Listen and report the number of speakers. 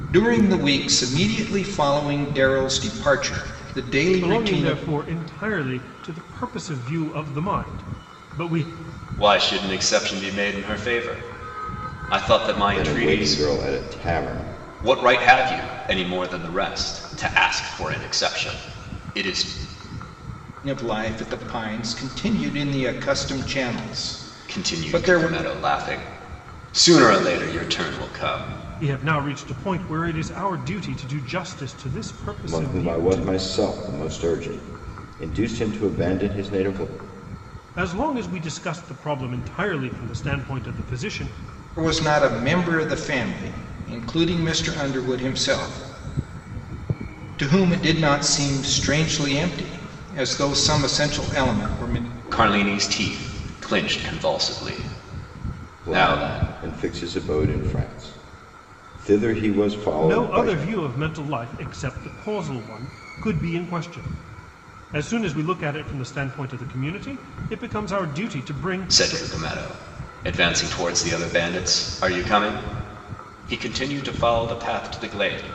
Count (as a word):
four